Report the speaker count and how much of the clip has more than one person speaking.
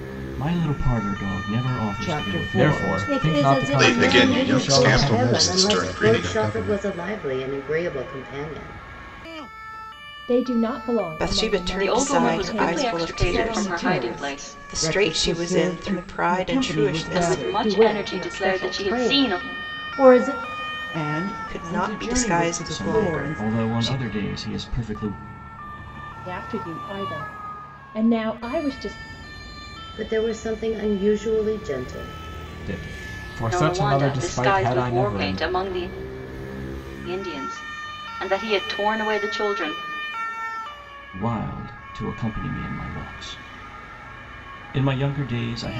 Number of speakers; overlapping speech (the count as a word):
ten, about 38%